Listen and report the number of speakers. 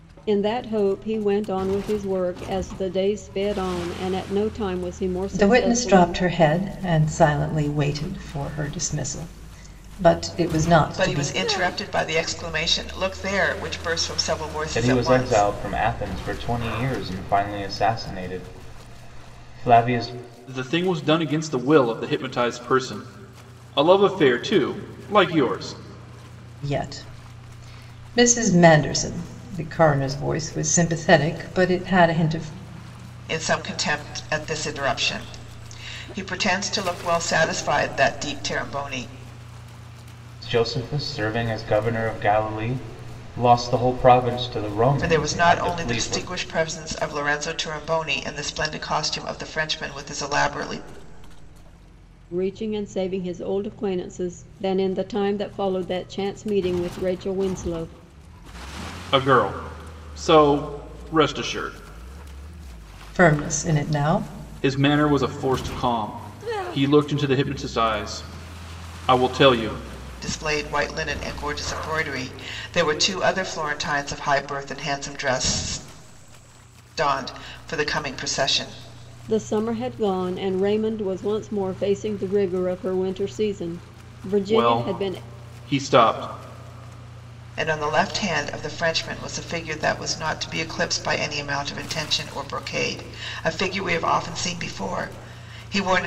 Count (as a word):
five